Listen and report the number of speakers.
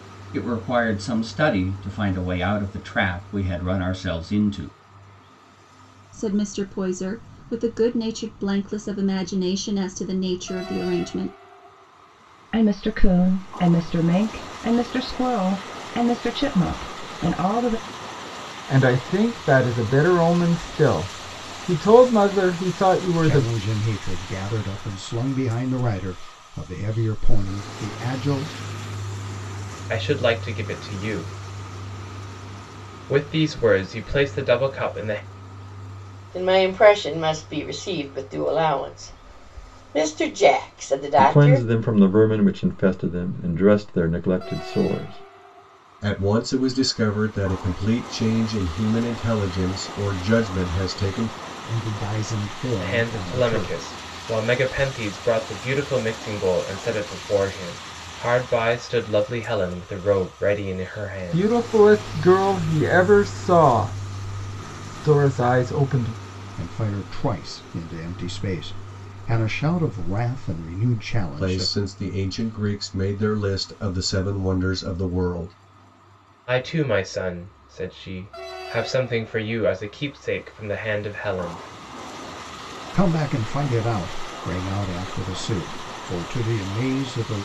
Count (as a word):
nine